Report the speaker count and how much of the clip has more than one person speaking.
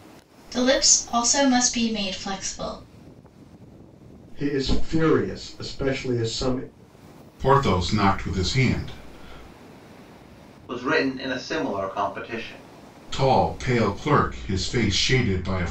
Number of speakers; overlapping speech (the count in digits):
4, no overlap